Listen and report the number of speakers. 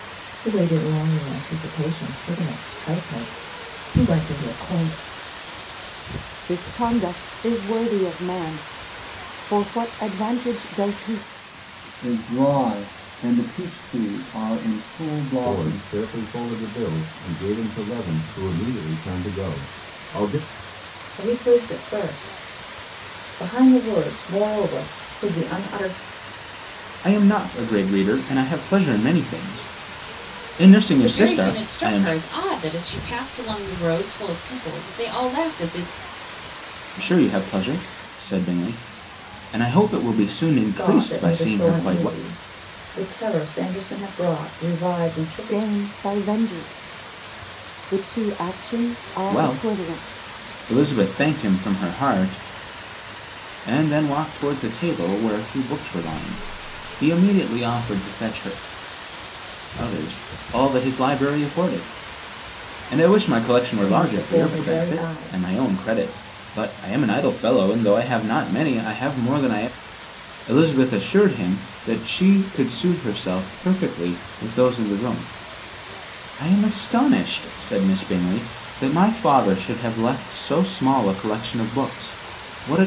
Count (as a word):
seven